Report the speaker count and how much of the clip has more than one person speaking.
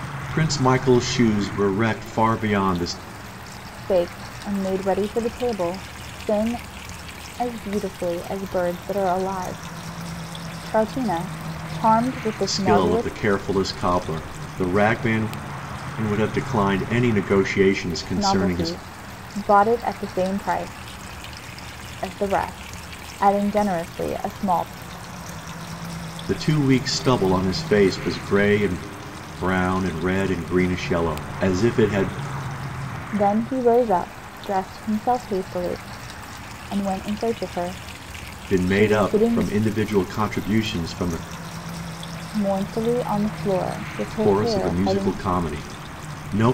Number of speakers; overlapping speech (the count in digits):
2, about 7%